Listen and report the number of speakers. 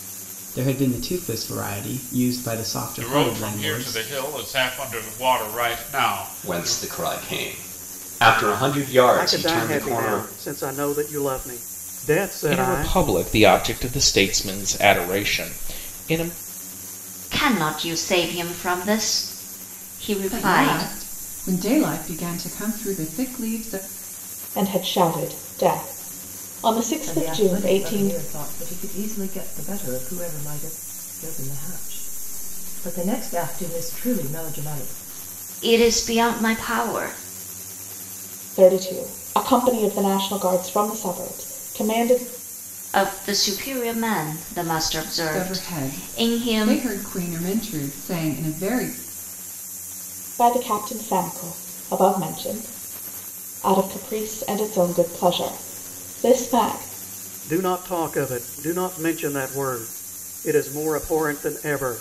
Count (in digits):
9